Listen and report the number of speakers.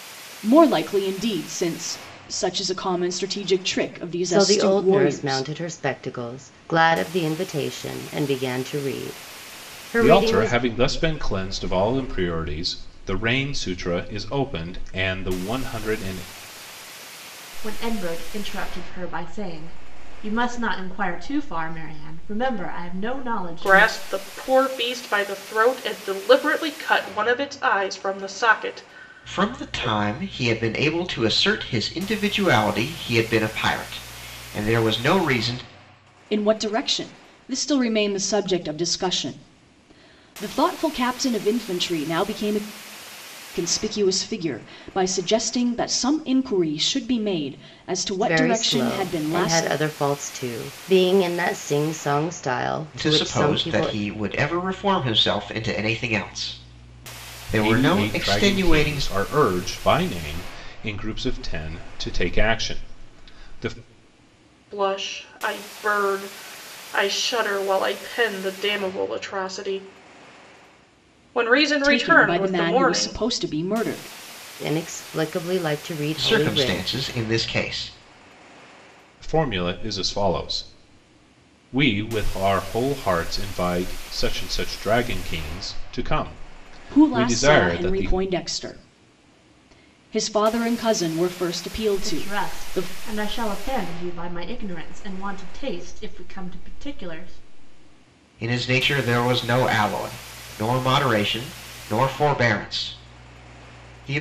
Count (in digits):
6